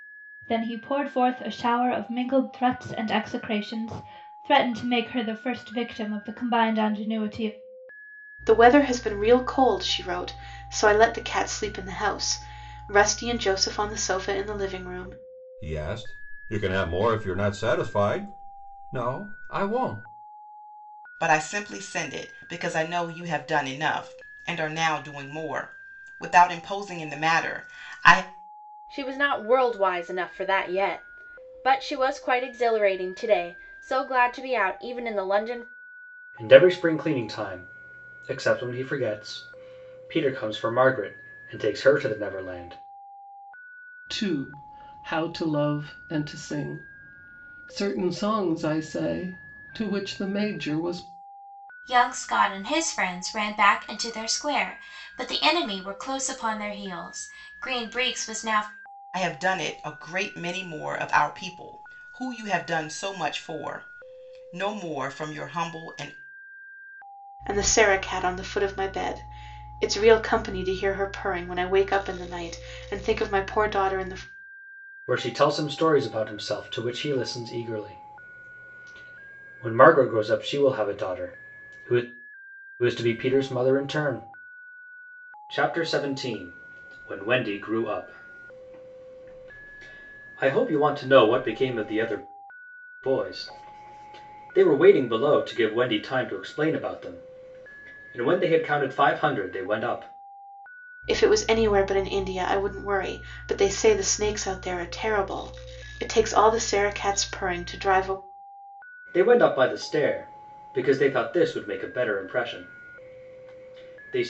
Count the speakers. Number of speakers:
8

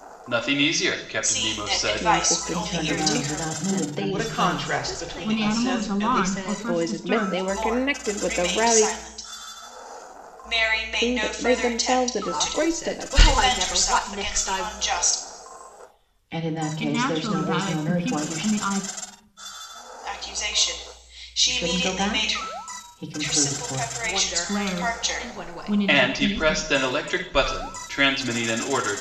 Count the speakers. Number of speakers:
7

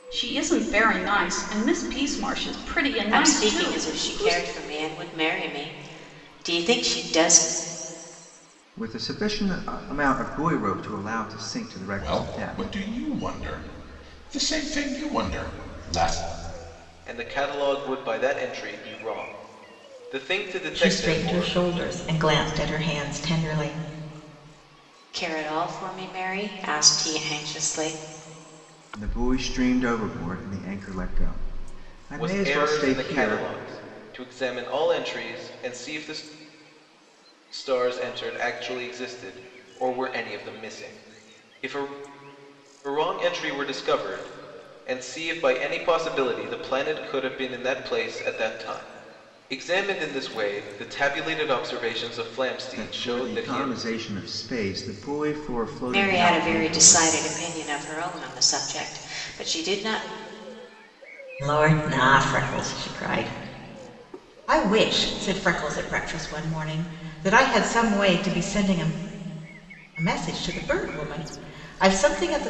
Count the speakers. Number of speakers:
6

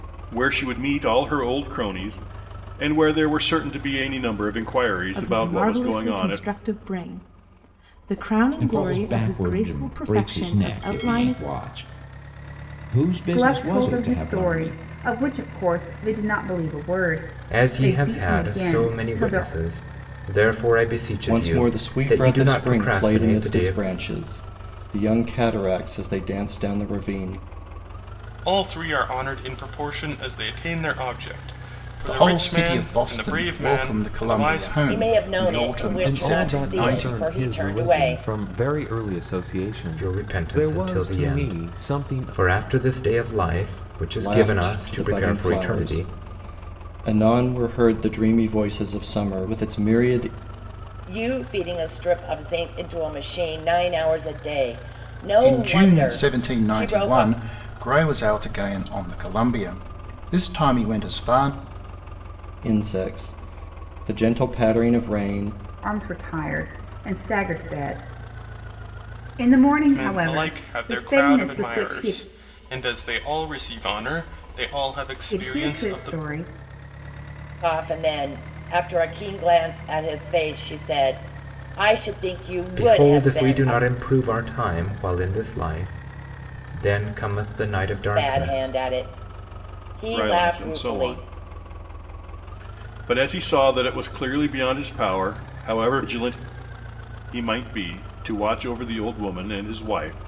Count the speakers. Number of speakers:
10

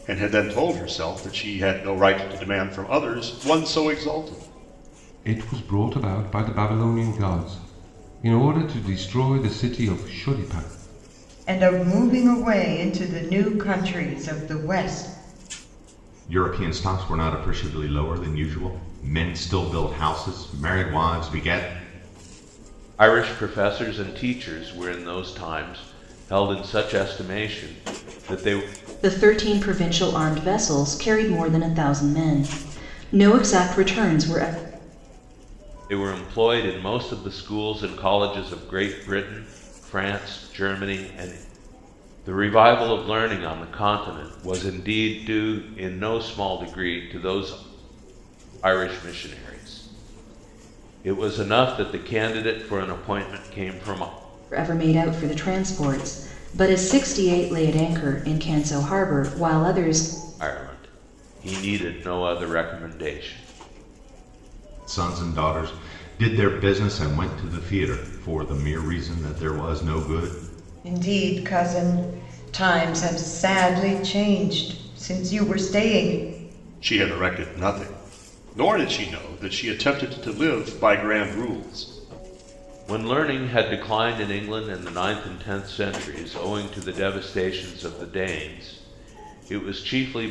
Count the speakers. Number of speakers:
6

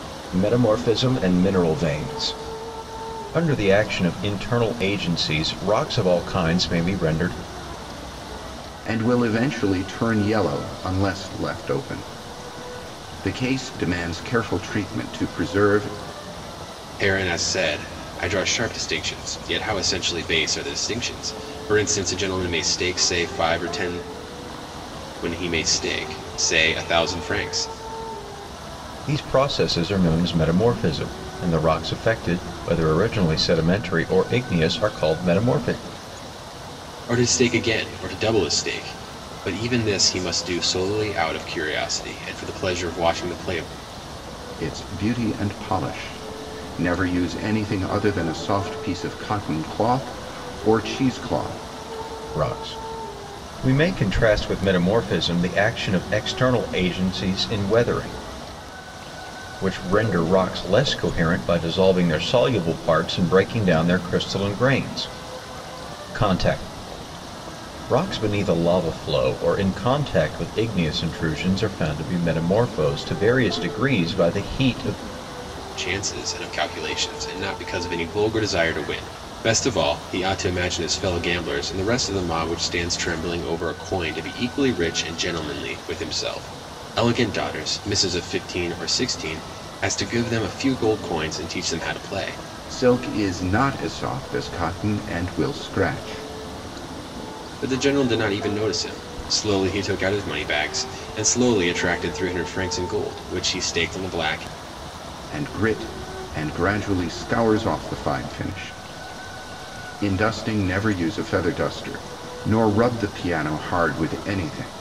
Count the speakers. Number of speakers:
3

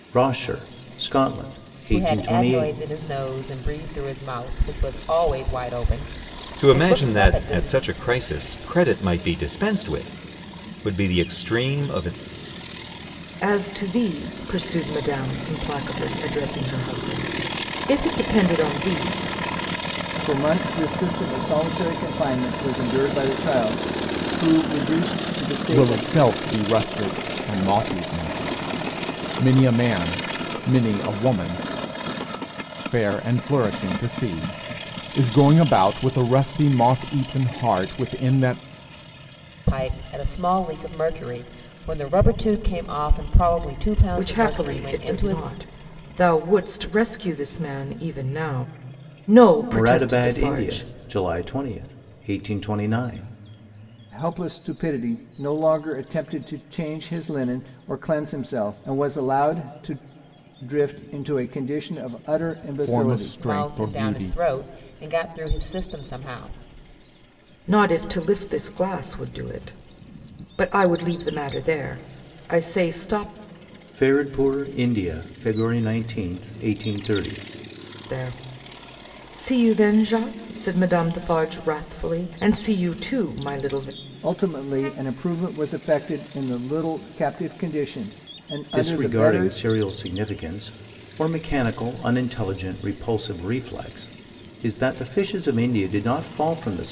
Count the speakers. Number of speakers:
6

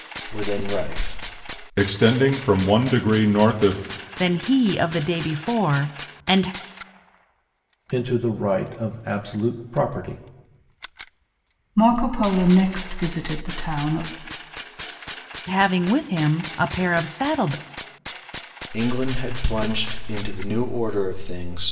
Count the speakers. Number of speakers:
5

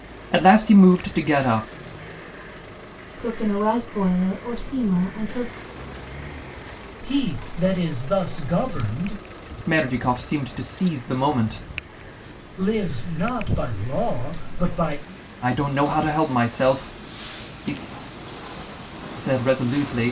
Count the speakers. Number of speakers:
3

